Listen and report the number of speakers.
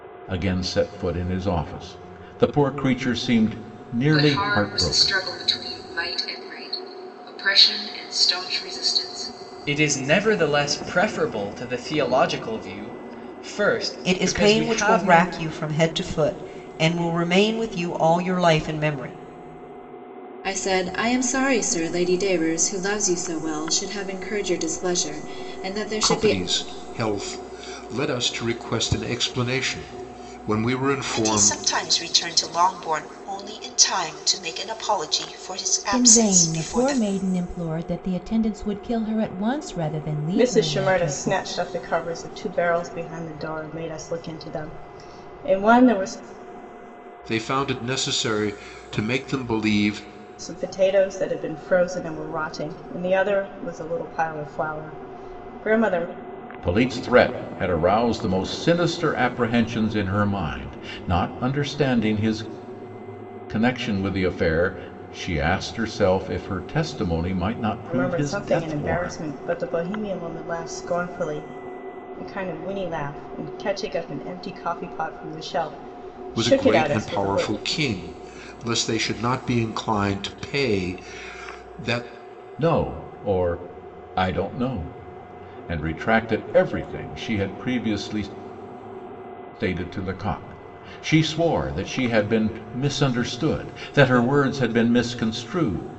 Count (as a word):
nine